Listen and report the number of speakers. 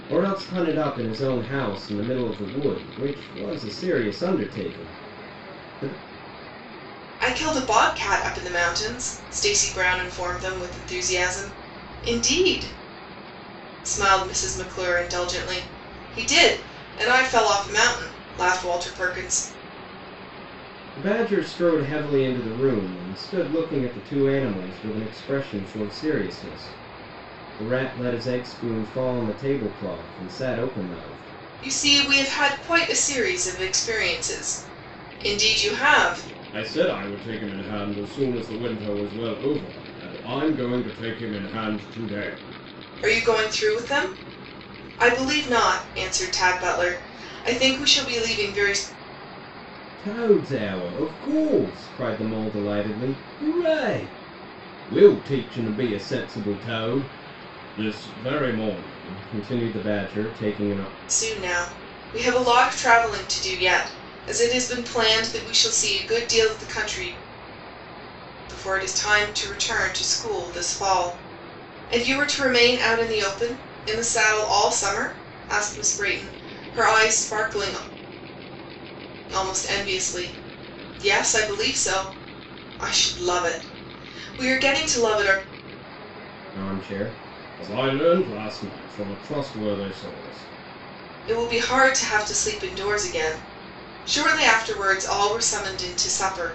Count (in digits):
2